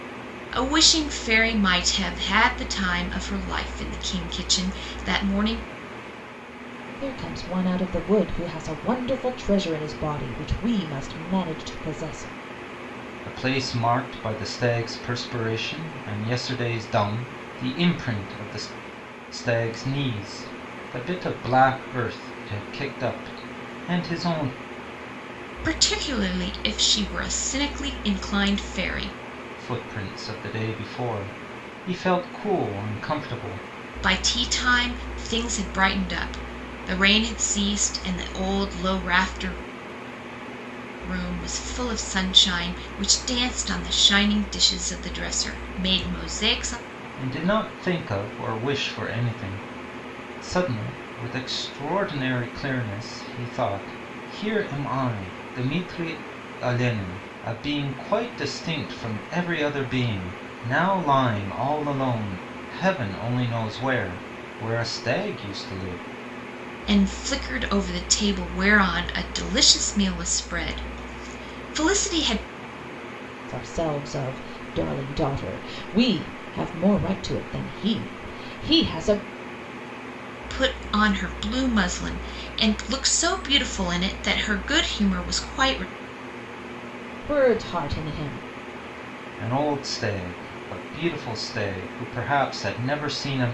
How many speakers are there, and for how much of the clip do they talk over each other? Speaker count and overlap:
three, no overlap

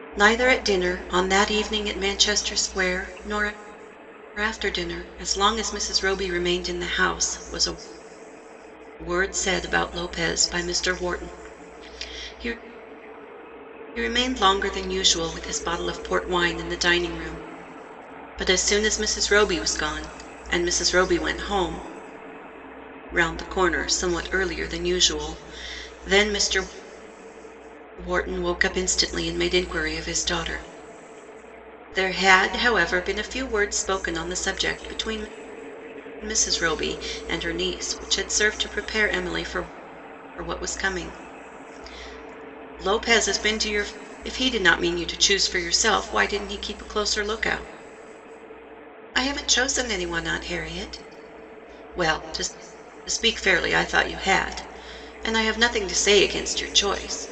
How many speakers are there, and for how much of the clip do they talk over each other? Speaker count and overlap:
one, no overlap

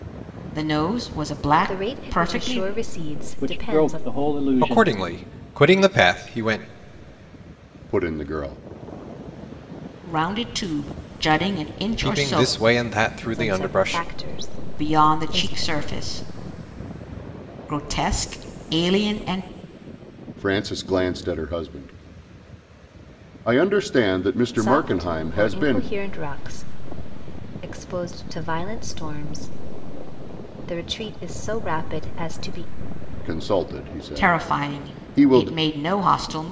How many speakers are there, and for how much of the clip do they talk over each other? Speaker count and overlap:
five, about 19%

